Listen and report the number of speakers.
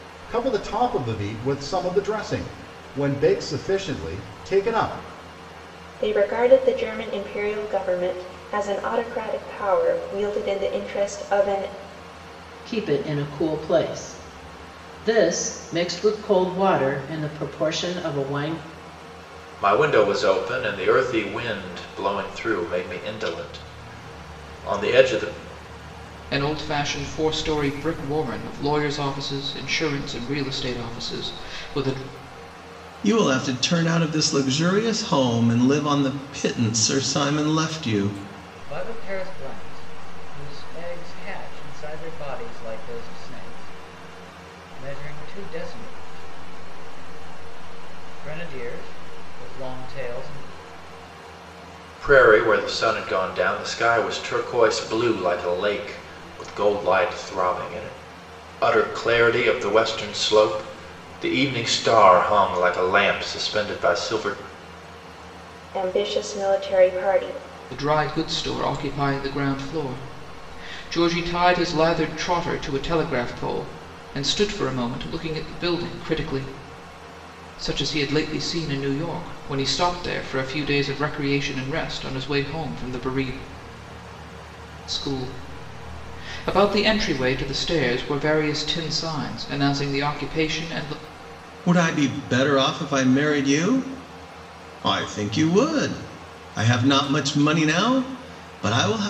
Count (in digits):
7